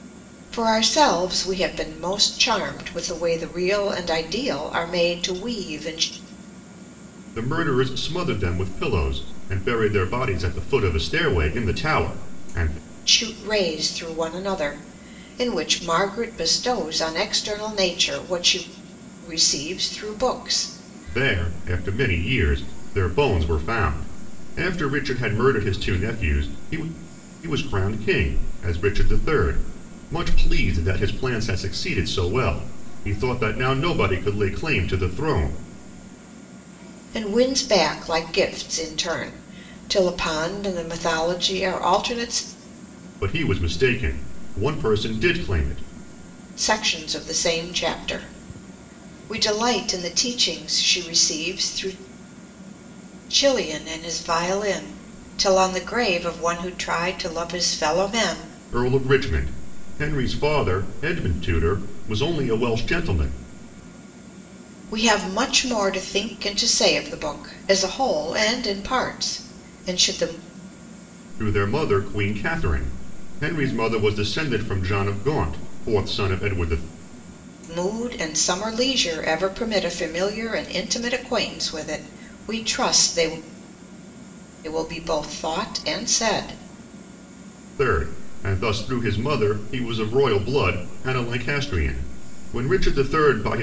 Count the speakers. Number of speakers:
two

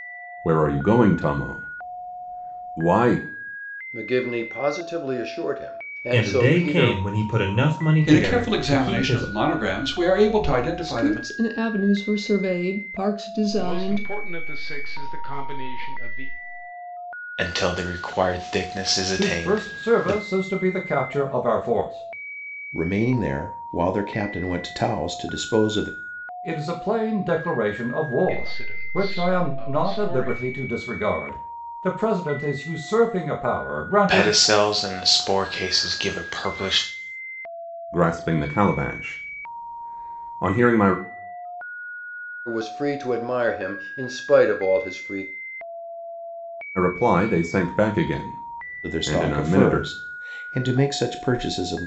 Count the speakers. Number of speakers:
nine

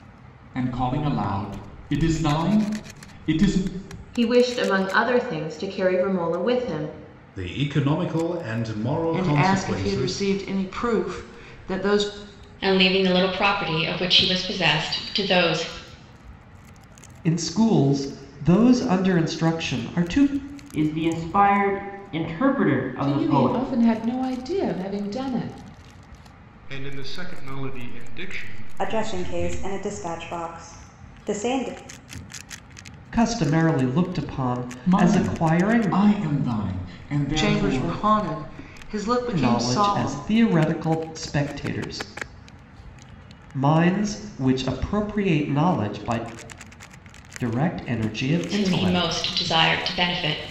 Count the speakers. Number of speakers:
ten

